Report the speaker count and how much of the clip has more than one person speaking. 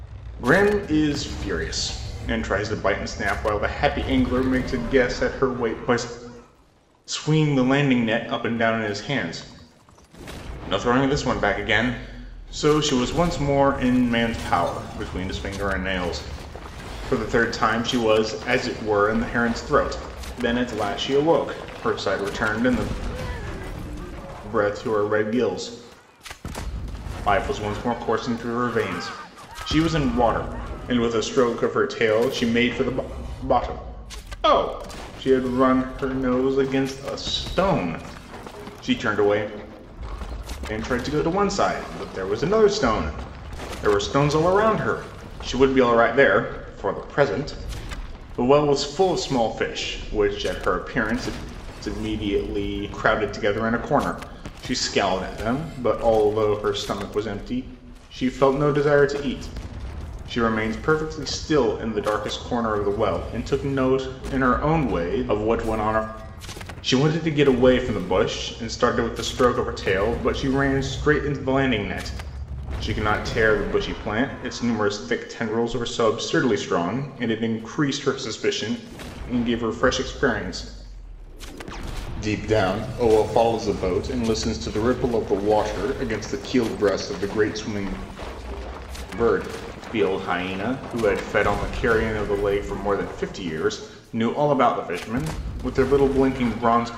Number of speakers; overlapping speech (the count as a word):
one, no overlap